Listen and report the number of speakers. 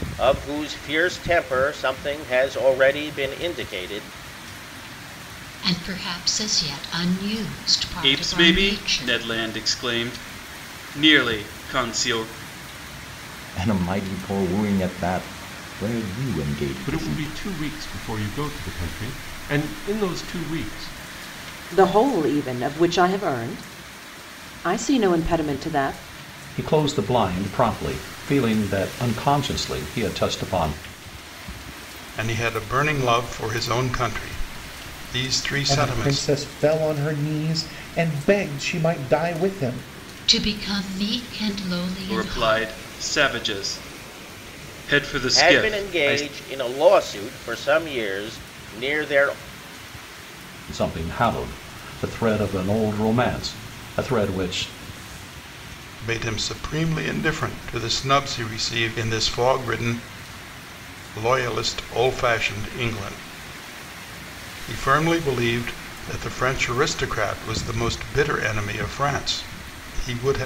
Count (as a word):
nine